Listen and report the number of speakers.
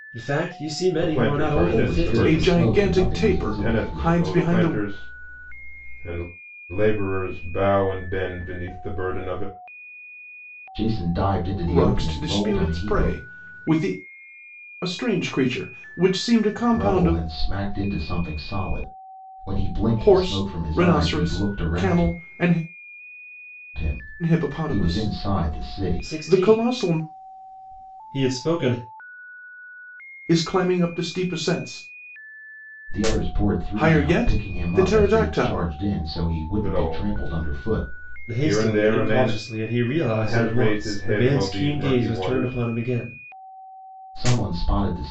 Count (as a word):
four